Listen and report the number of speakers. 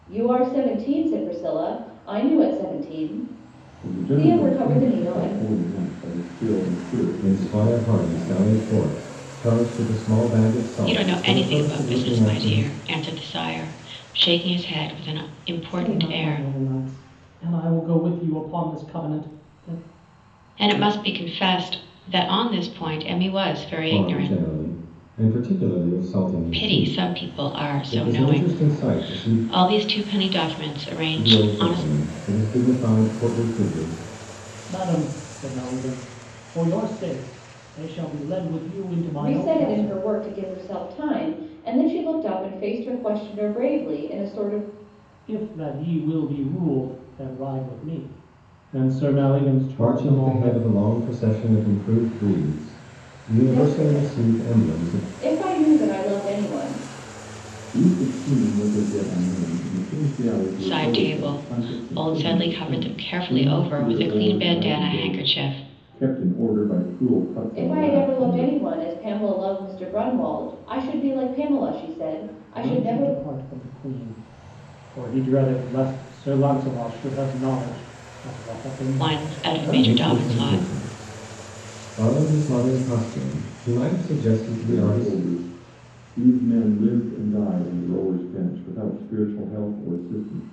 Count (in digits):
5